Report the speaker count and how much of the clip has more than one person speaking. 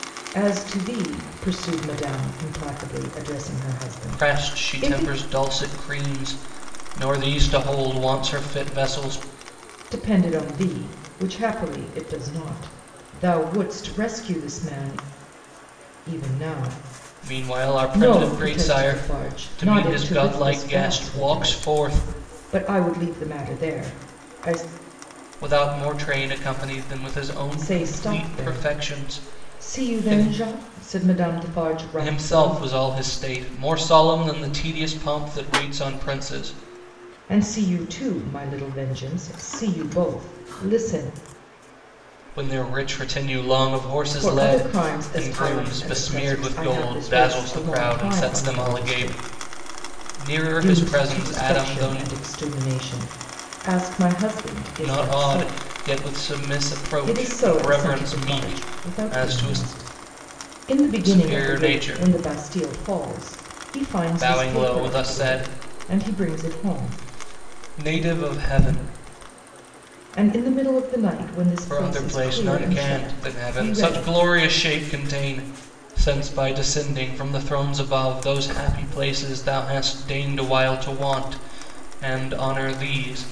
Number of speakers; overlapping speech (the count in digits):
2, about 31%